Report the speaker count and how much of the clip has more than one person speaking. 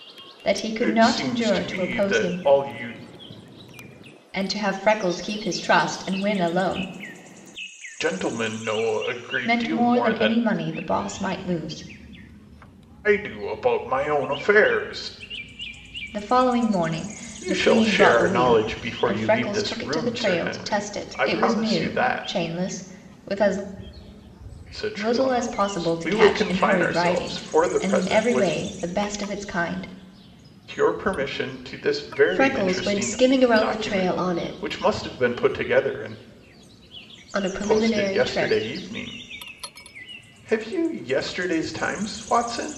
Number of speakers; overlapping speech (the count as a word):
two, about 32%